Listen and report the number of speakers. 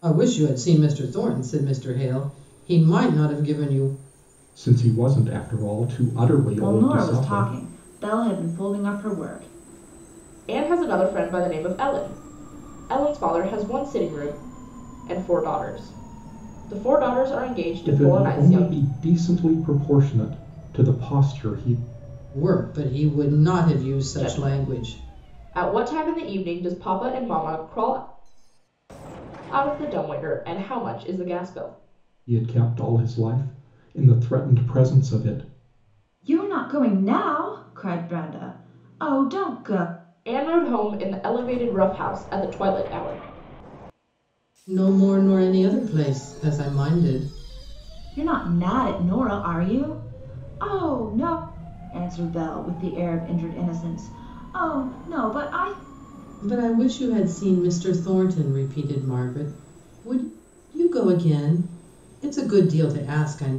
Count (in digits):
4